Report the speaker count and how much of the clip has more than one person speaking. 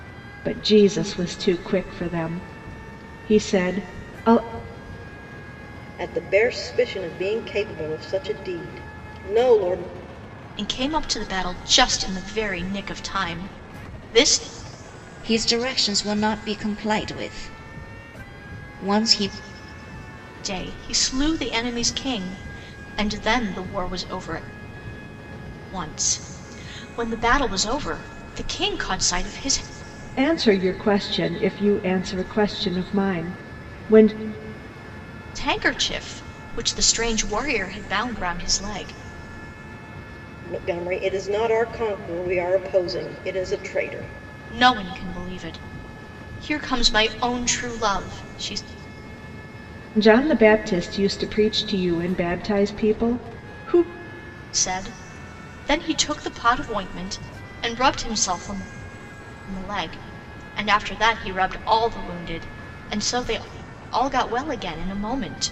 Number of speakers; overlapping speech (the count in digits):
4, no overlap